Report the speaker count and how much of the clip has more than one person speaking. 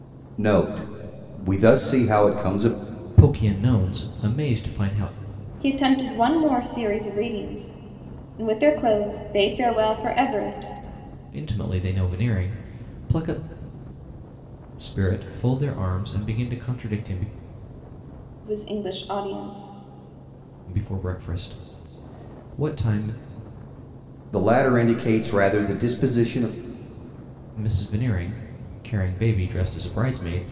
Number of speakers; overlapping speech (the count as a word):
three, no overlap